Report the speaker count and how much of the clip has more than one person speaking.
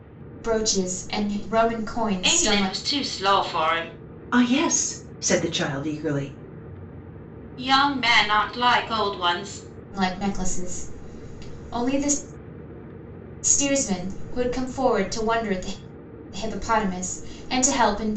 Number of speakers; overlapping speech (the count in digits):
3, about 3%